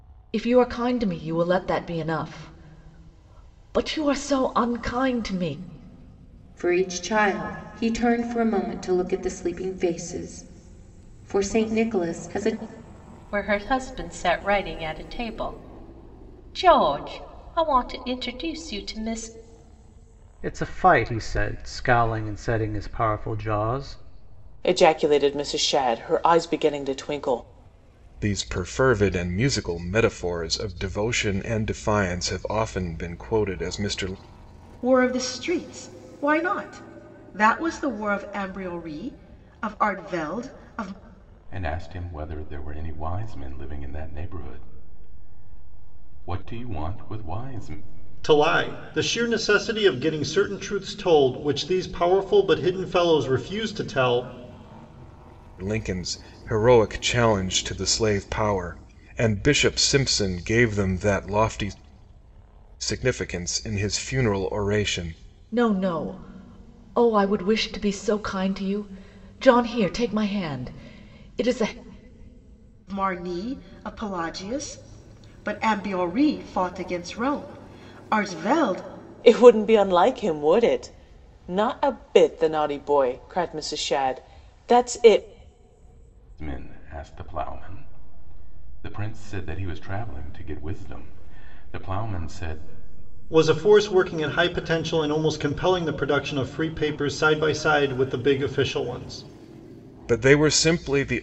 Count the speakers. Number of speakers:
9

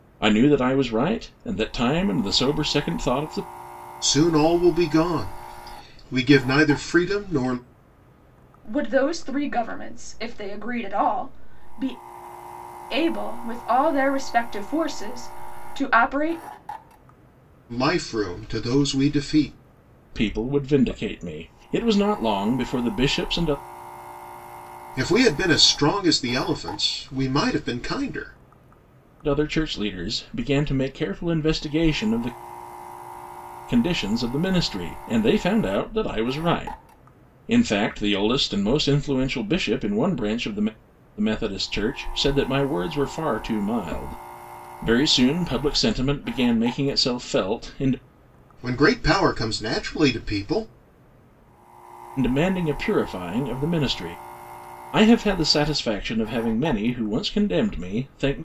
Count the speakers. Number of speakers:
3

